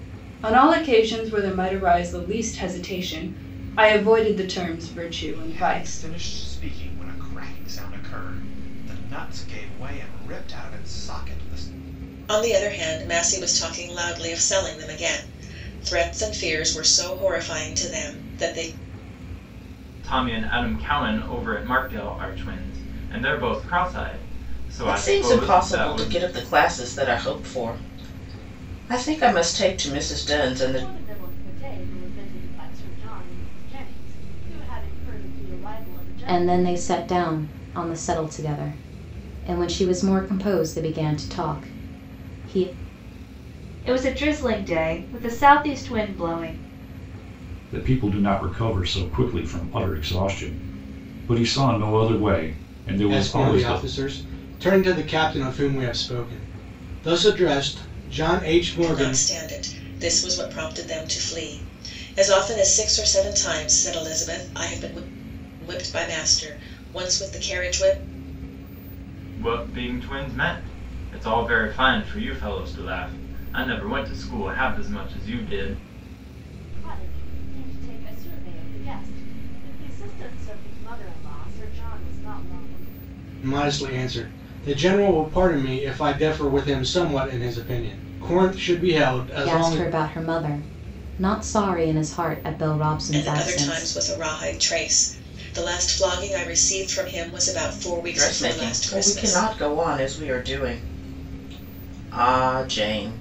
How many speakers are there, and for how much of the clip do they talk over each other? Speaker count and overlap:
10, about 7%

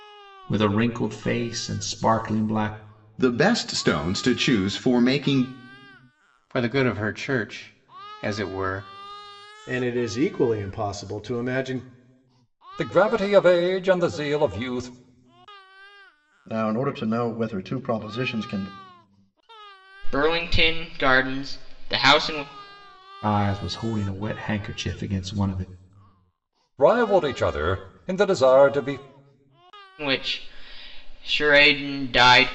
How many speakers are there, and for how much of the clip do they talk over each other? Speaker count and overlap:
7, no overlap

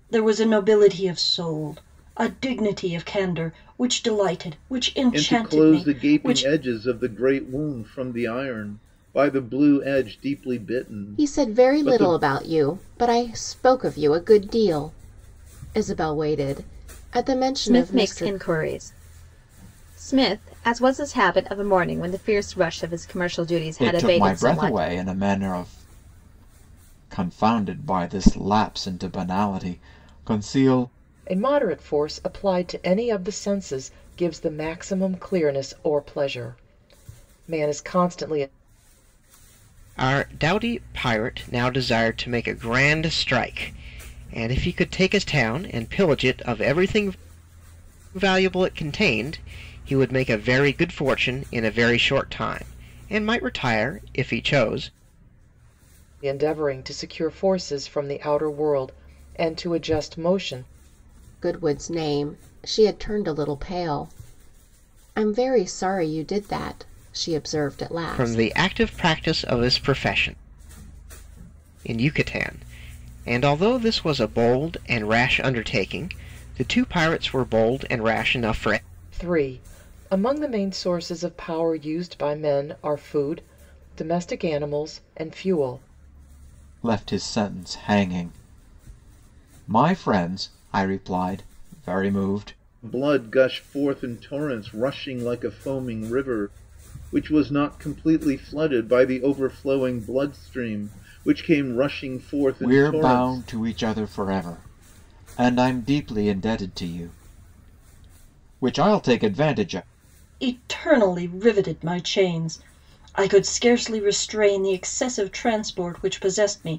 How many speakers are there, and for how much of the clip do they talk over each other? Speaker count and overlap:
7, about 5%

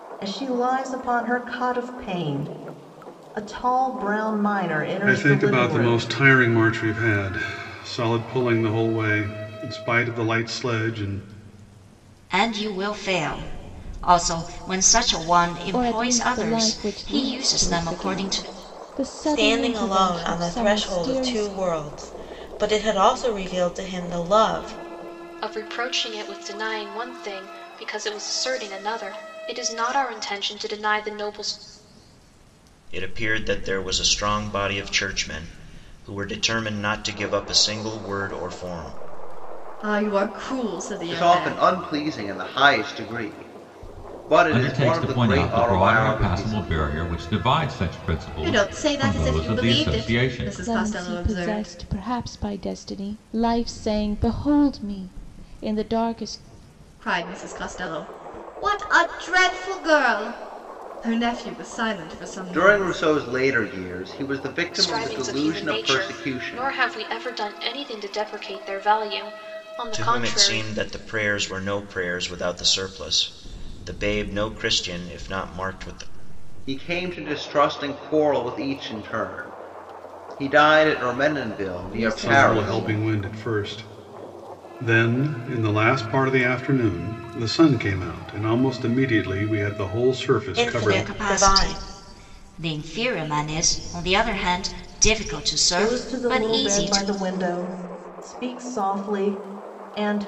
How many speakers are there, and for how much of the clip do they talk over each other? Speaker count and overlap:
10, about 20%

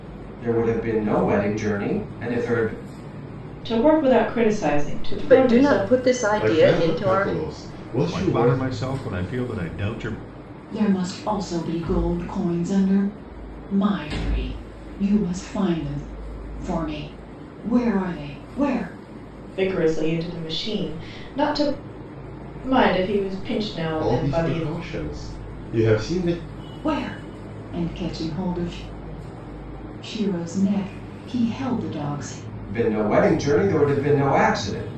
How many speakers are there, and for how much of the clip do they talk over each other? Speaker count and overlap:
6, about 9%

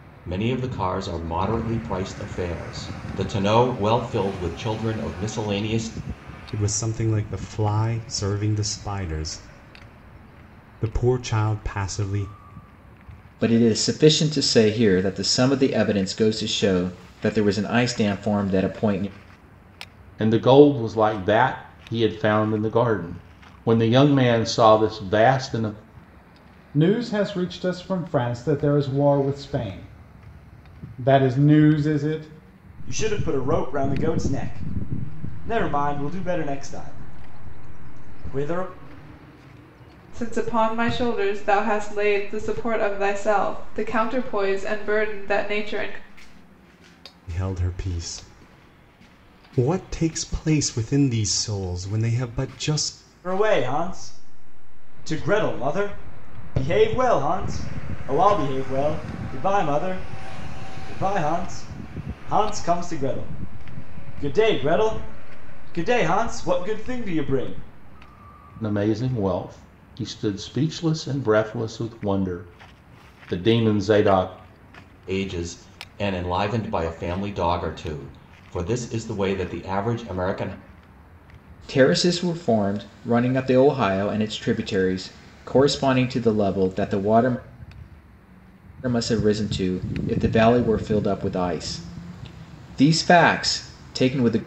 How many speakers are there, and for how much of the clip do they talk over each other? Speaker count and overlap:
7, no overlap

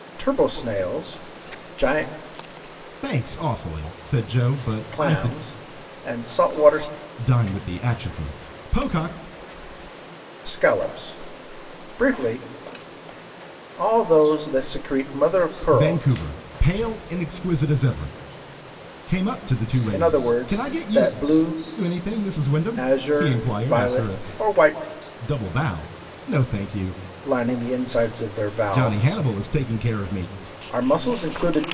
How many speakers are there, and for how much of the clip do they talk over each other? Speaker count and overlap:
2, about 13%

